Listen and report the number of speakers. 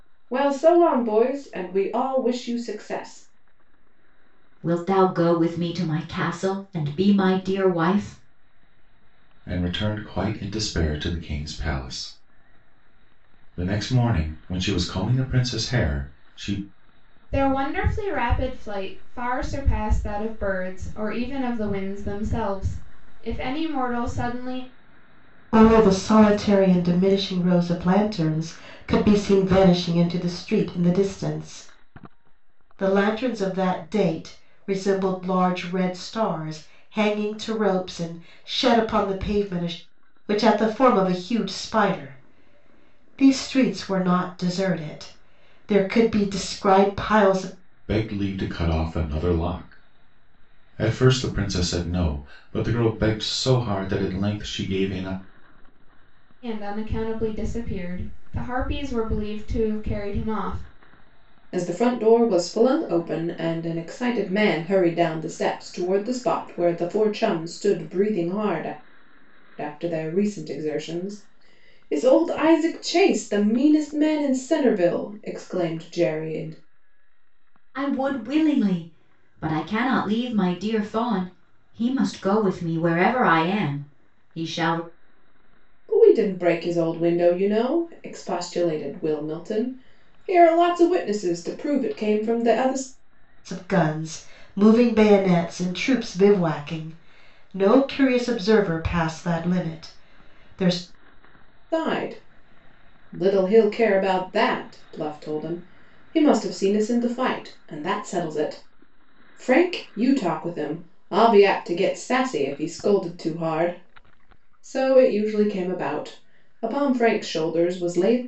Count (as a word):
five